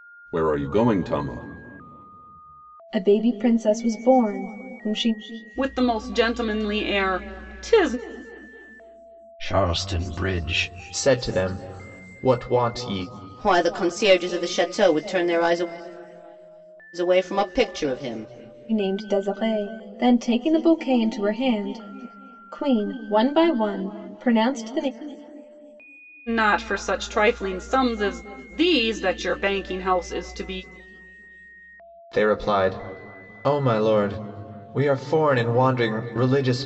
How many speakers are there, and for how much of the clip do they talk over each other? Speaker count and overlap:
6, no overlap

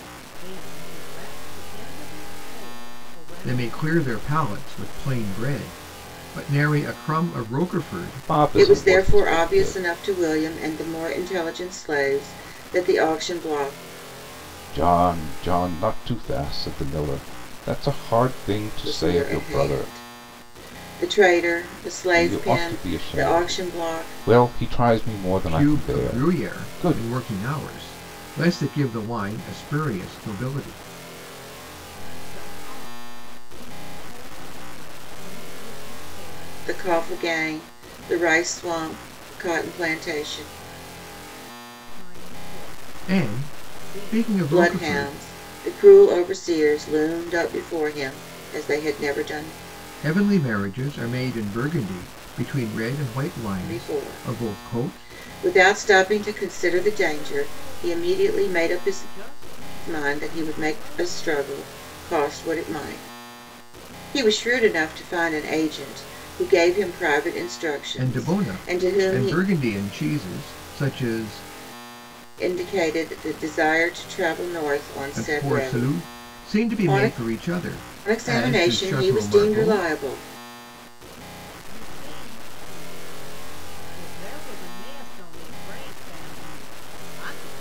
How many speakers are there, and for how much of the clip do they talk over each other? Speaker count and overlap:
4, about 25%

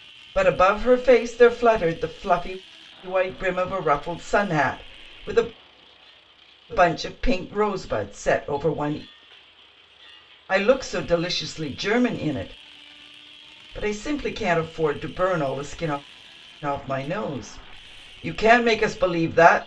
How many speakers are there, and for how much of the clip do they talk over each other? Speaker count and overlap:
1, no overlap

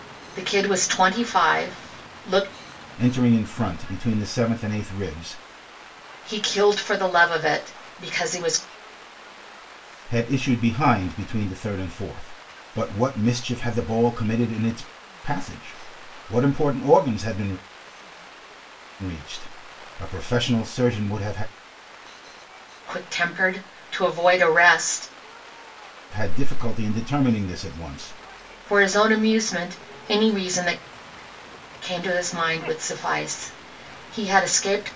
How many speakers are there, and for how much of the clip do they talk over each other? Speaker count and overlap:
2, no overlap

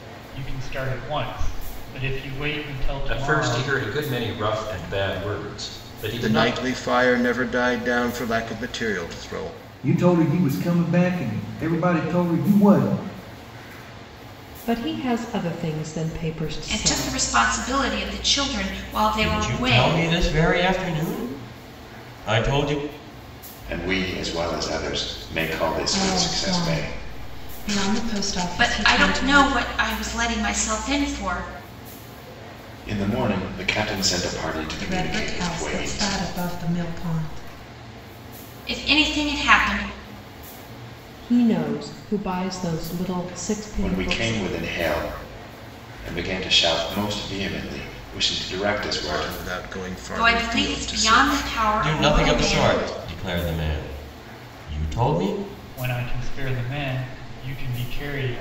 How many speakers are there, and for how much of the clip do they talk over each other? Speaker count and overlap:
9, about 16%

